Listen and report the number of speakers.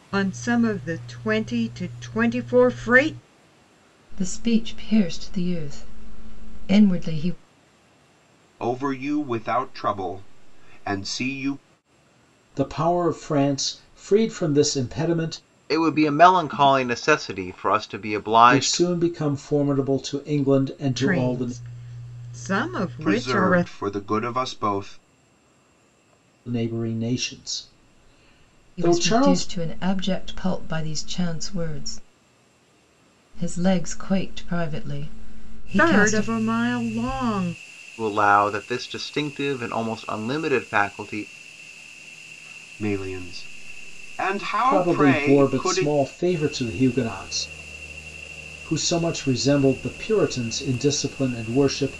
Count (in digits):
5